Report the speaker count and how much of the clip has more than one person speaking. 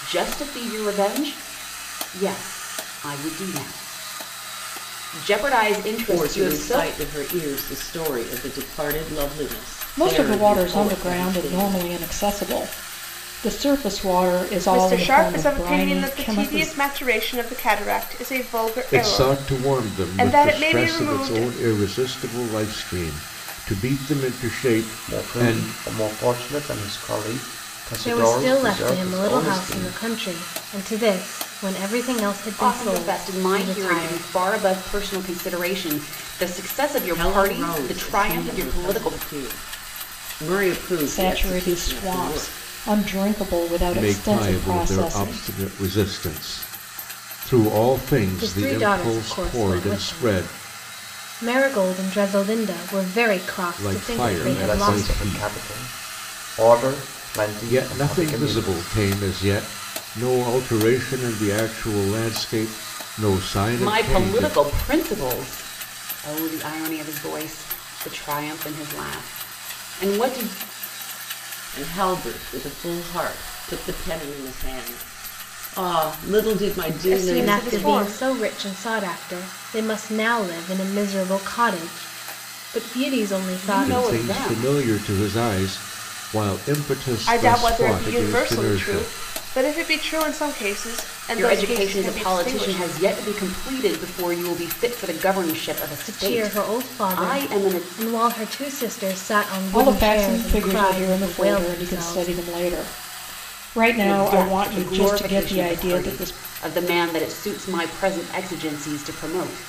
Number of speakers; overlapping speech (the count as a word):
seven, about 33%